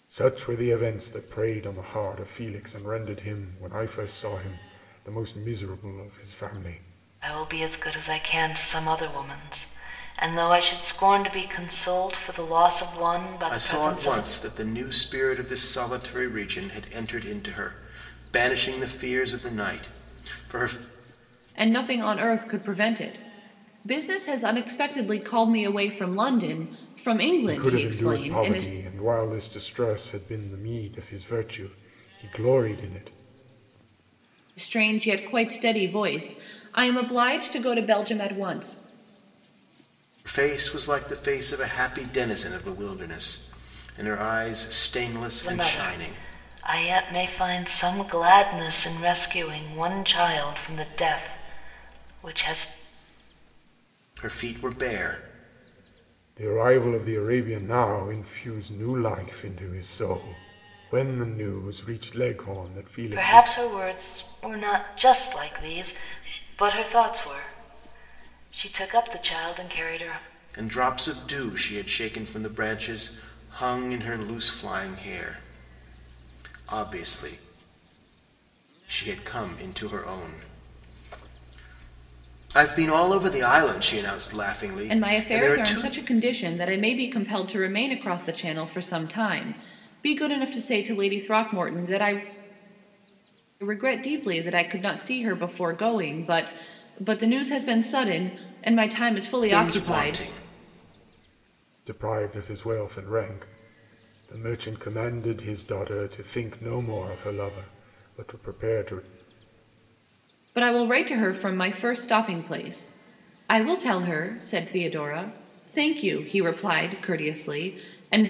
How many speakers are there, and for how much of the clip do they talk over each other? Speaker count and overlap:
4, about 5%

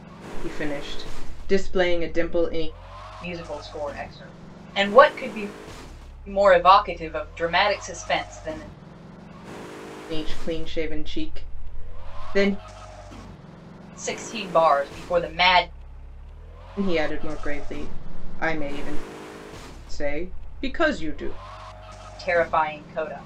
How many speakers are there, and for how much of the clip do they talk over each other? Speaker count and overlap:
2, no overlap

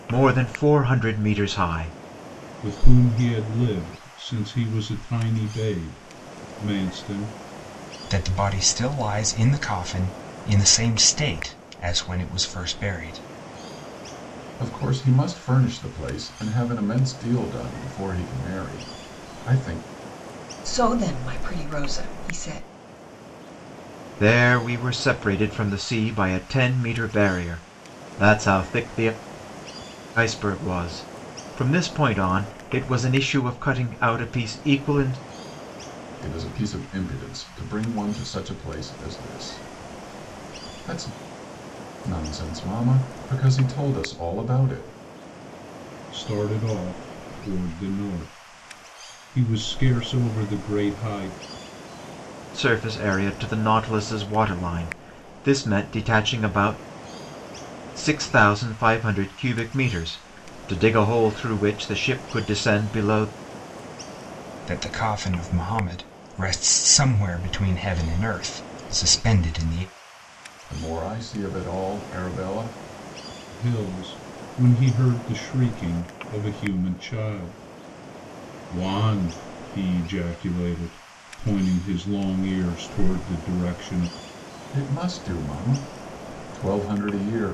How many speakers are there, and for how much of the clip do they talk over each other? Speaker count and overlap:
5, no overlap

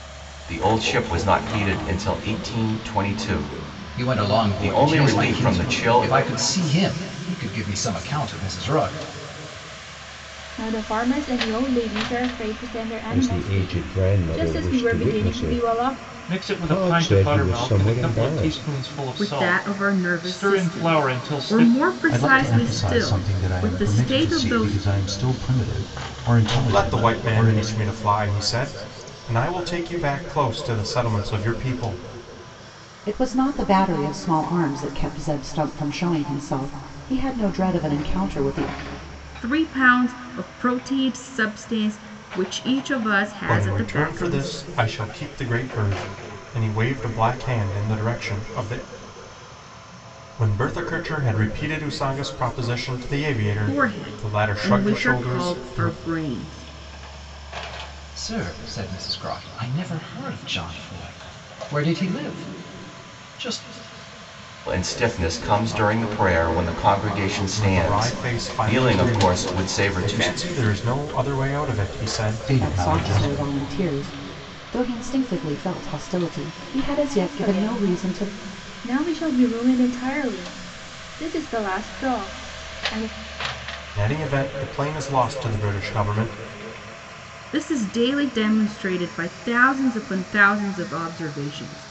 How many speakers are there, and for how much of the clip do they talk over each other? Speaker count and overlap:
9, about 25%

